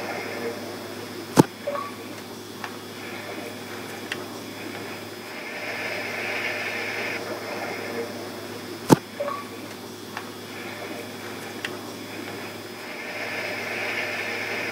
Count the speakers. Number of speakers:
zero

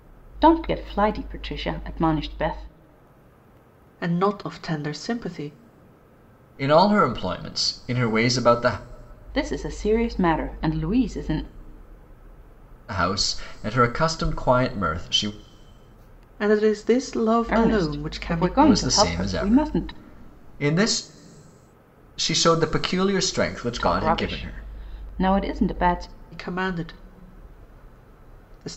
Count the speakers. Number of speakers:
three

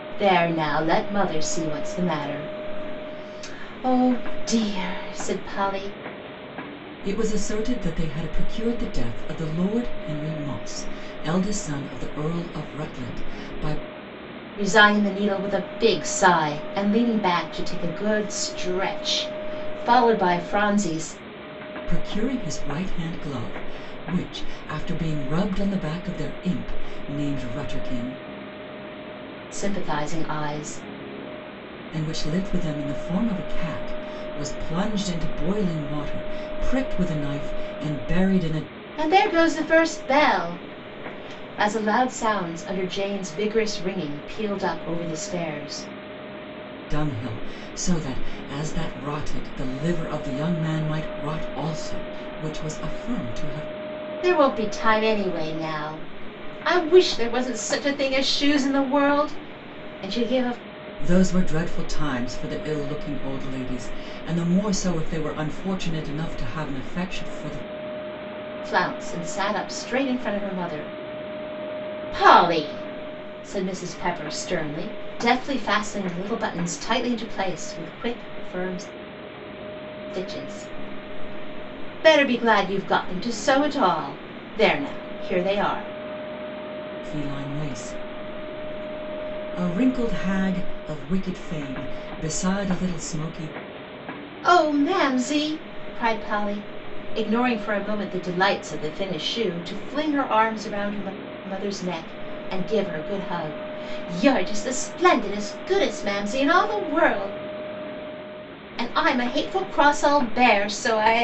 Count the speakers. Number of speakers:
two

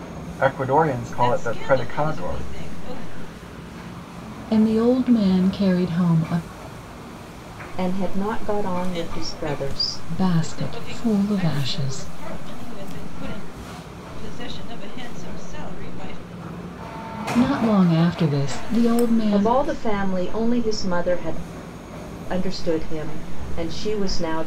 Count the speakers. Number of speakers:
four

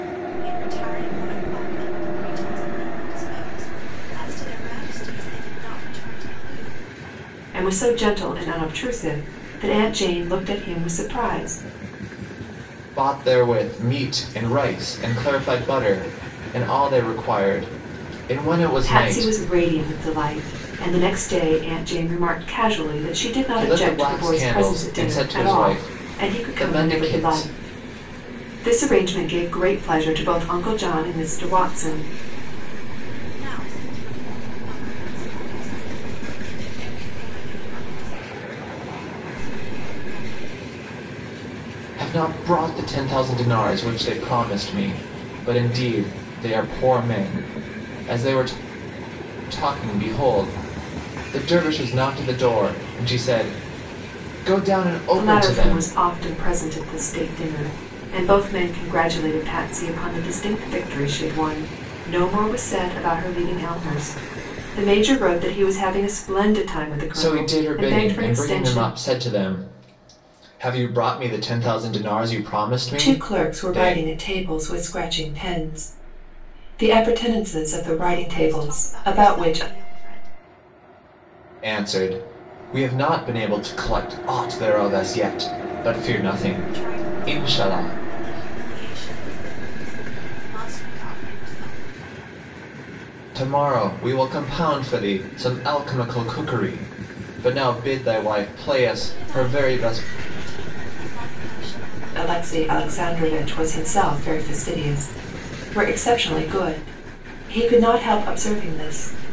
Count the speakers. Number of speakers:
three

